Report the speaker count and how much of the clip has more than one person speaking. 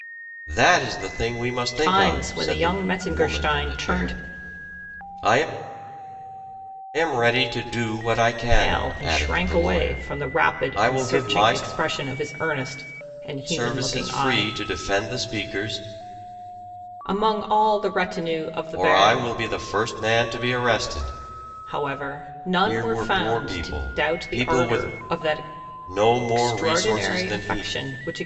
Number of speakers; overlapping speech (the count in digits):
2, about 38%